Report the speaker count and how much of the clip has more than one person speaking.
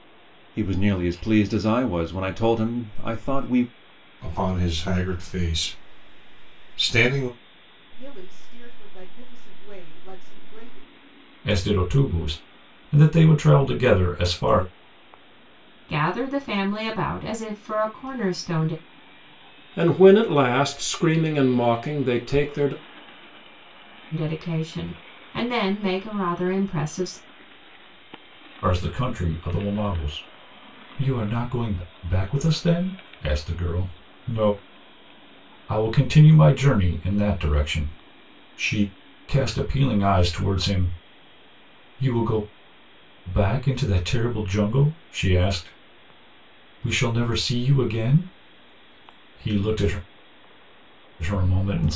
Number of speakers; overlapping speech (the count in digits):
6, no overlap